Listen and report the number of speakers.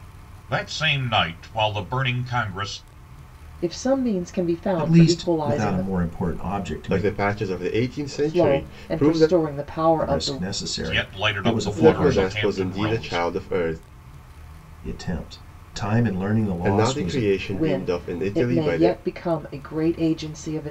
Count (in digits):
4